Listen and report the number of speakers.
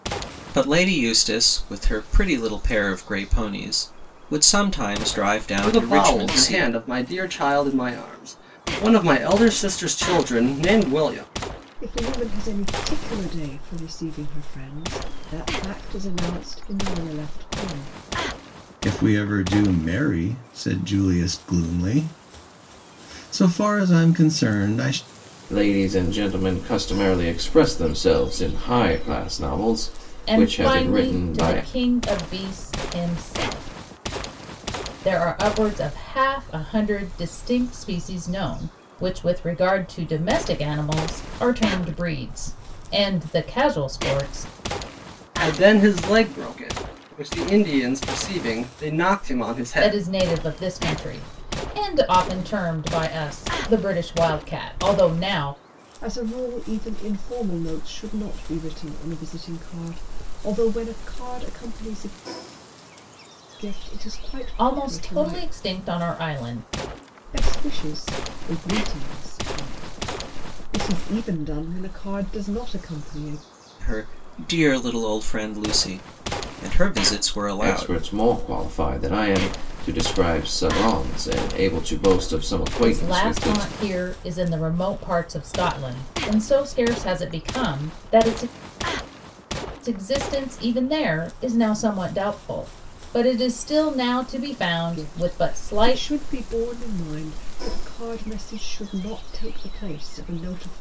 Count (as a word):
six